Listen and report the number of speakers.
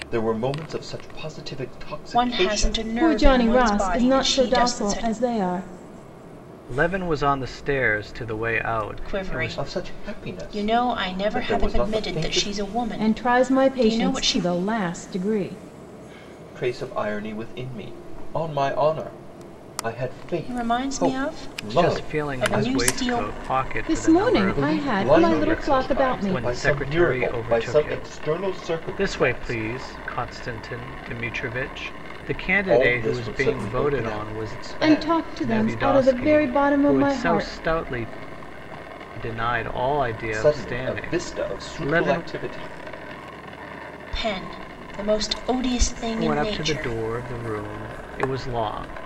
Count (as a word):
four